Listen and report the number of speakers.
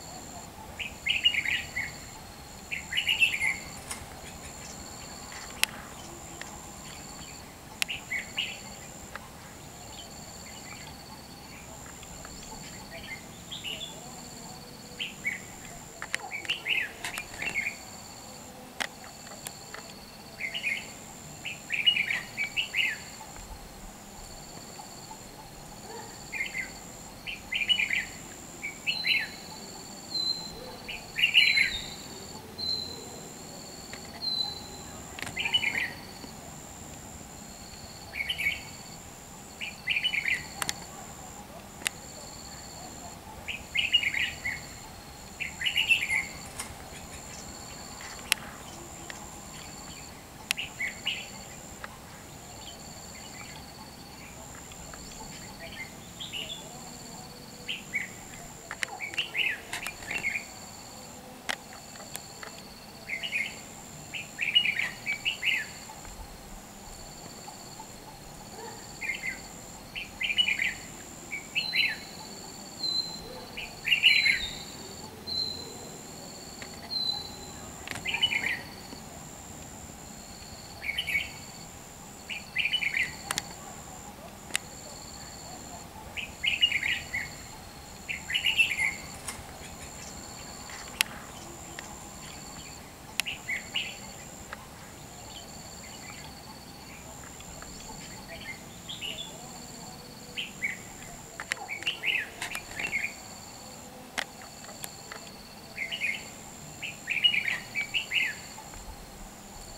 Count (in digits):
0